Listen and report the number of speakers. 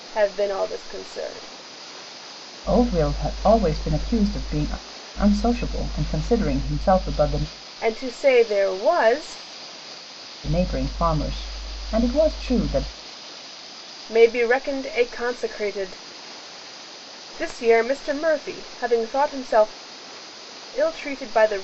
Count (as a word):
two